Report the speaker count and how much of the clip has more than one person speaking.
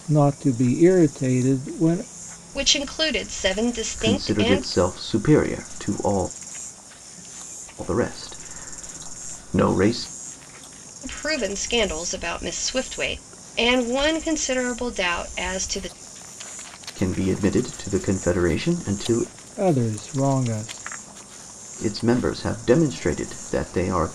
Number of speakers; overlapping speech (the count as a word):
three, about 3%